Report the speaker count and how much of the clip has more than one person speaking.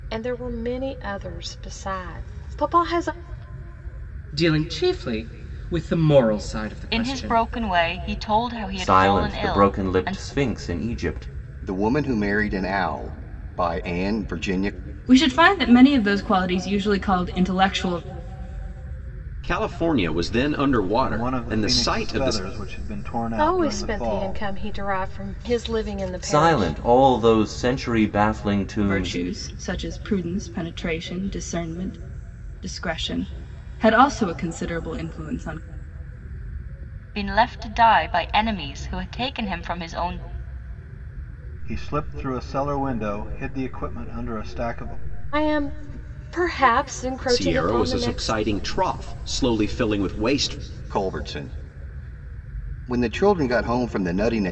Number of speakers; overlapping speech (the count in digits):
8, about 12%